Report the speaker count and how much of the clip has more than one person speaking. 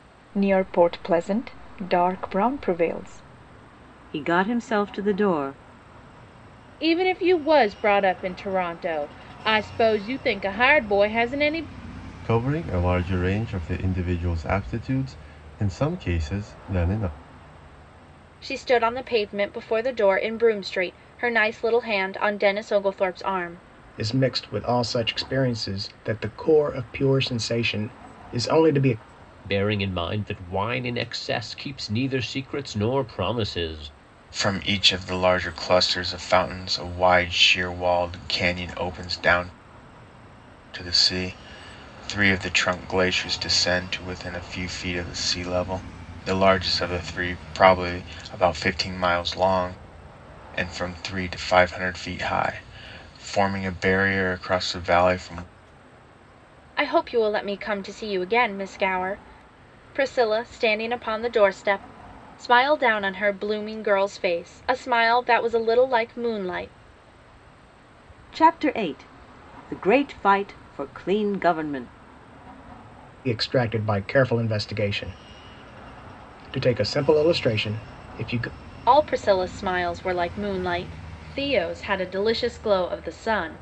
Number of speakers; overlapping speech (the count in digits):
8, no overlap